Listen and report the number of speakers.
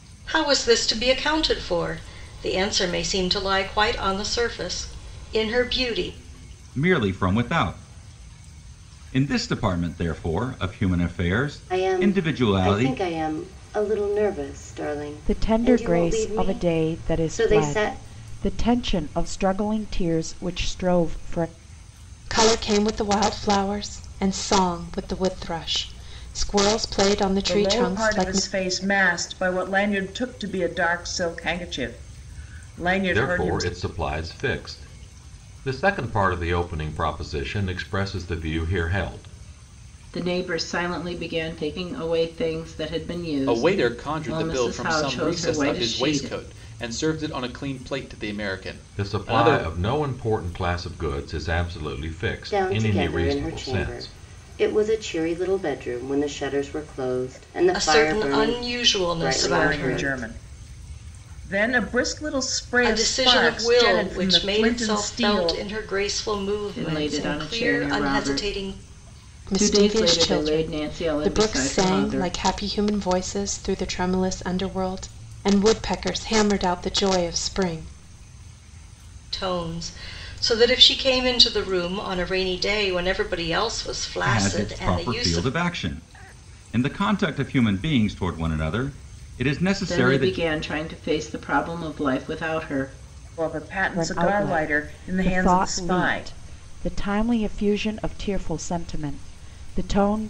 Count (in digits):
9